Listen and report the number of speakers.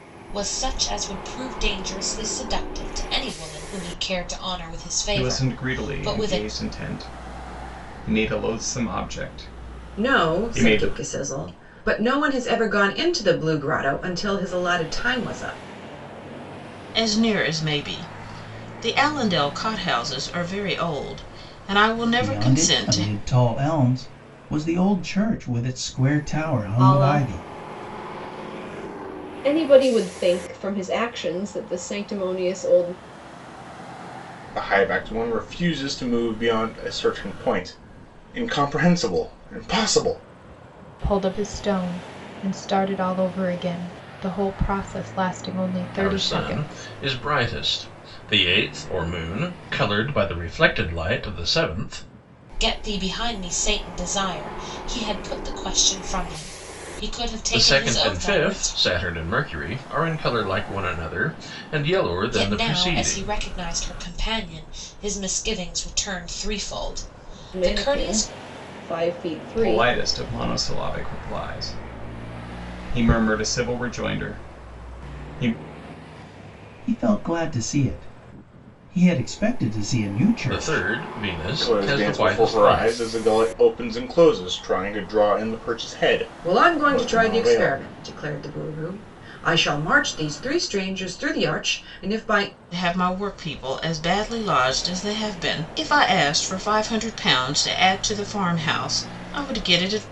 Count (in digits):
9